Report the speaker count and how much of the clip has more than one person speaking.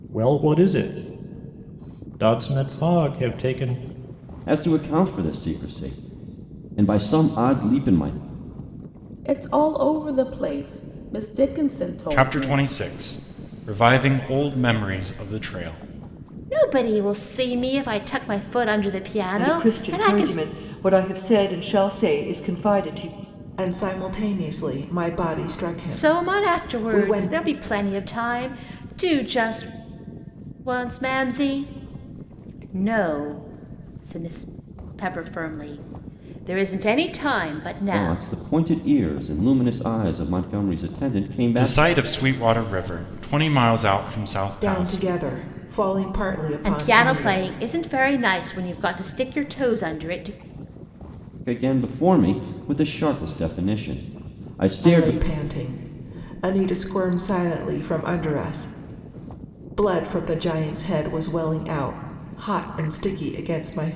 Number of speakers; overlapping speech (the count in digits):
7, about 9%